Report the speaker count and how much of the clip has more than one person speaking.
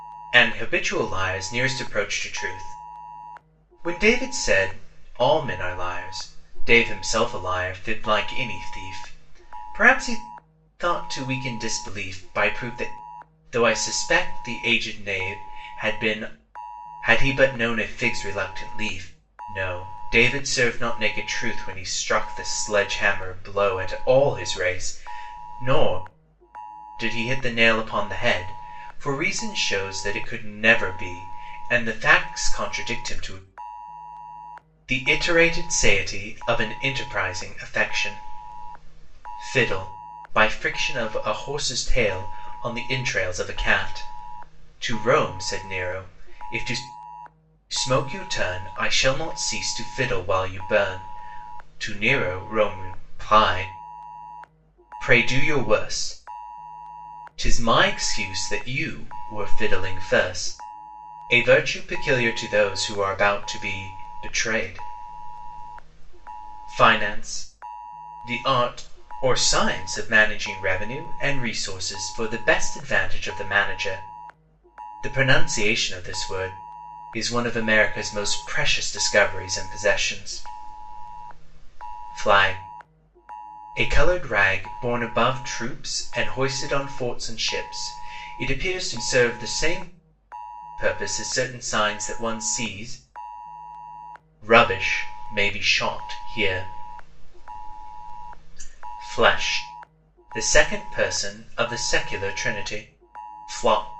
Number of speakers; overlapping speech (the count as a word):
one, no overlap